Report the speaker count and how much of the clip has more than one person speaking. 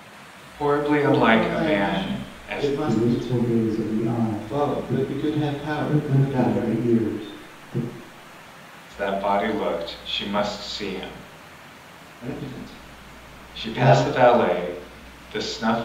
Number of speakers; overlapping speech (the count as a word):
three, about 29%